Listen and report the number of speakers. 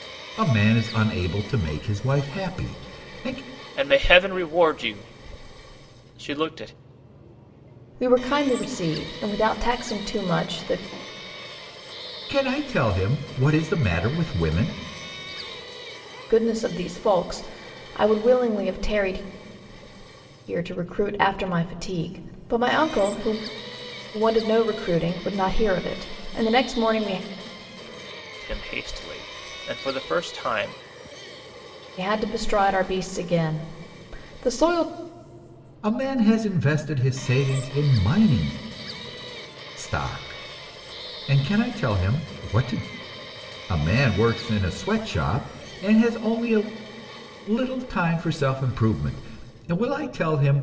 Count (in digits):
3